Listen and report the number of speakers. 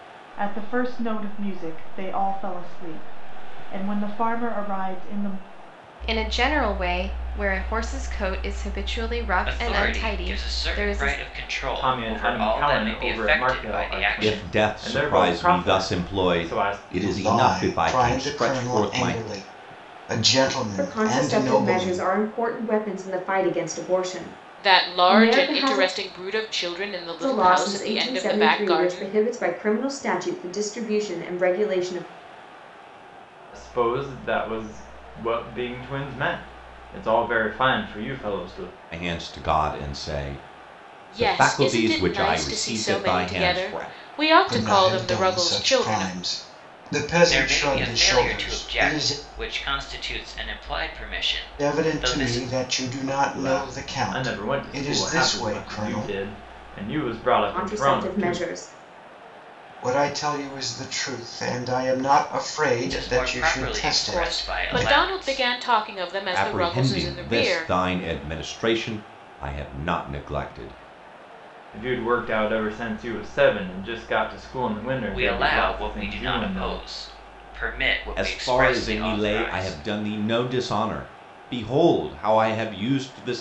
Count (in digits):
8